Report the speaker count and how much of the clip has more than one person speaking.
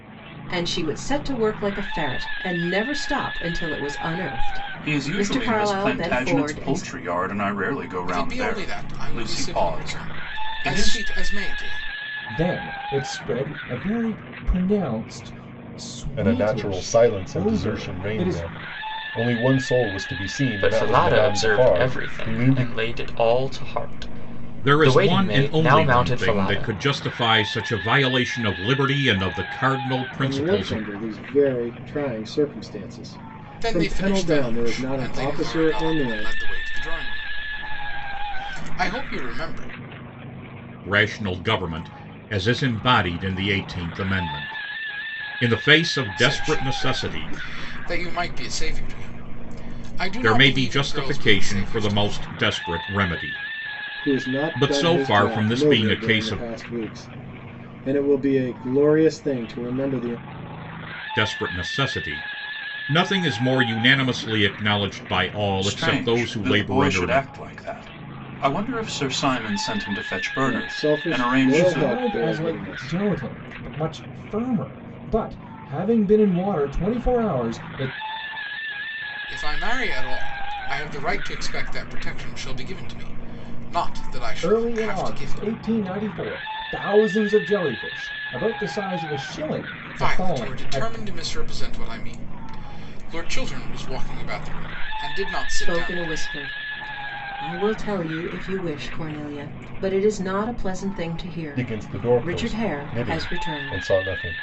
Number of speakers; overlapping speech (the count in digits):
8, about 29%